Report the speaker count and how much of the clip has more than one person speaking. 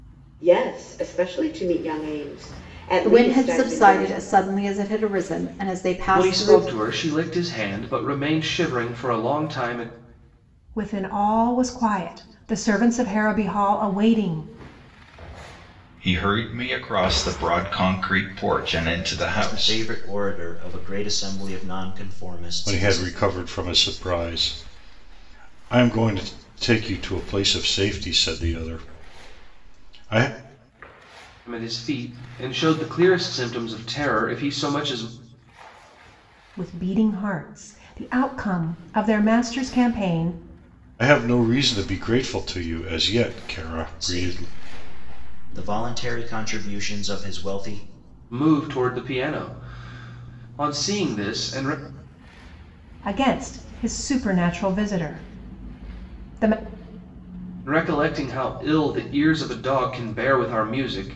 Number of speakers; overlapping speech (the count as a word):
seven, about 5%